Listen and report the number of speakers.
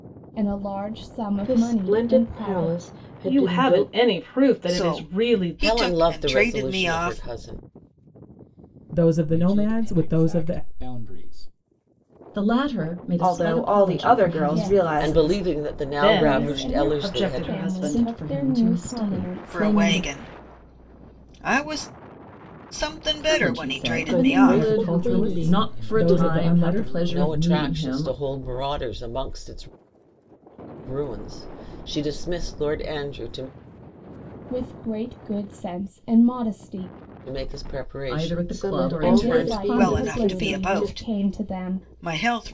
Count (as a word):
nine